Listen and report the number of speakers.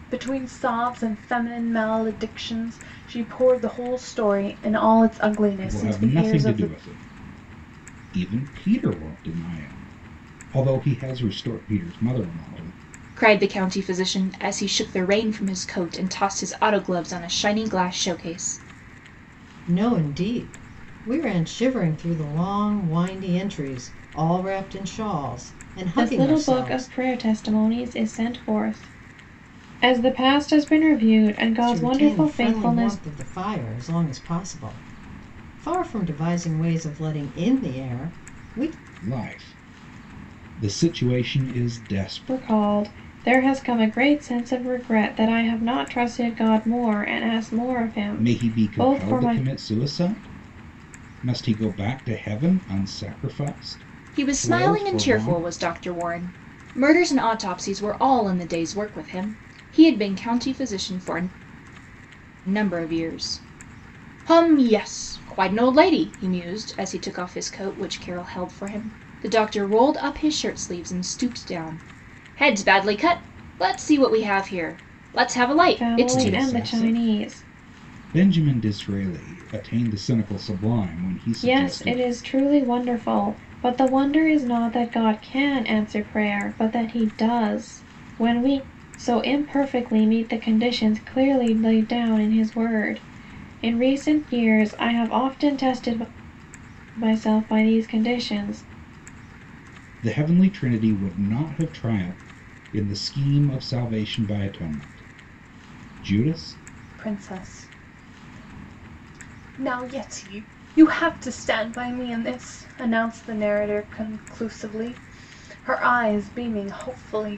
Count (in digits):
5